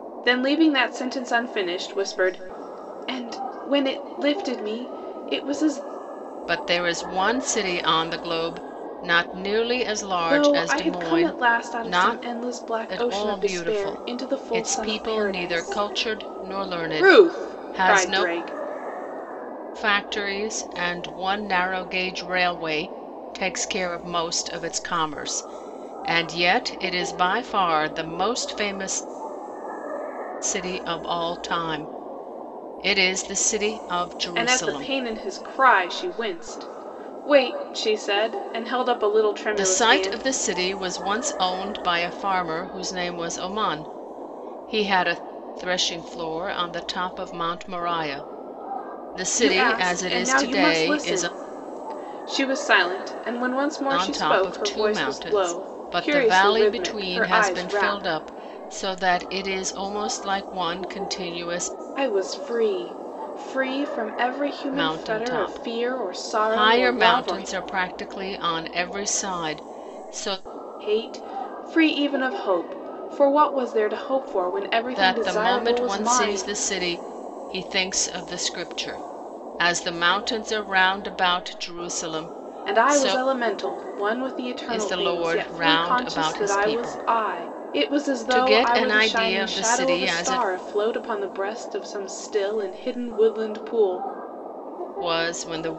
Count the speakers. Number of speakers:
2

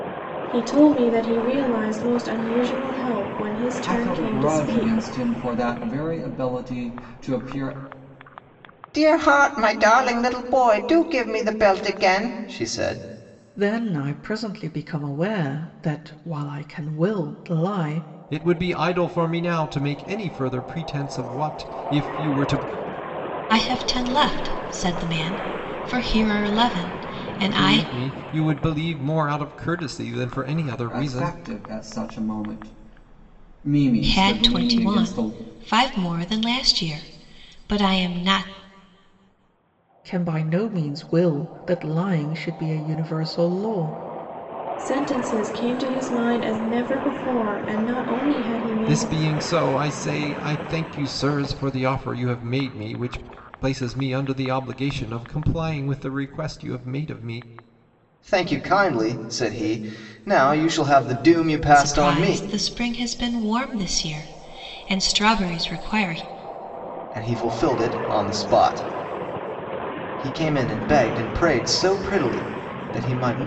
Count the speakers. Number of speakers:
6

